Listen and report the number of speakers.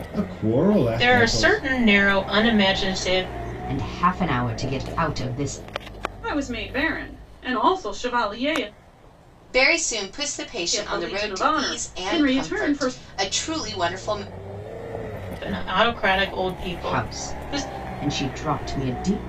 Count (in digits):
5